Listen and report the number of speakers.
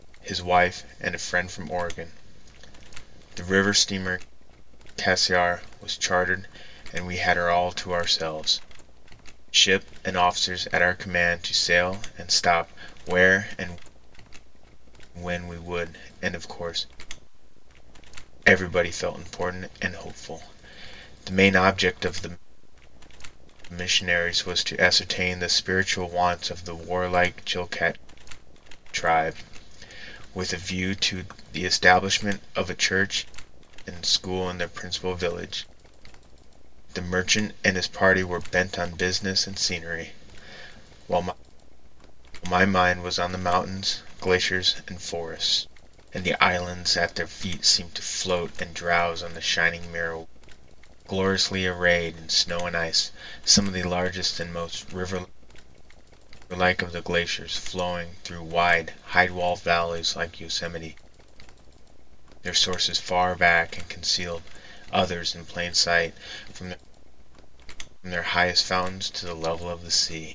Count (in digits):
1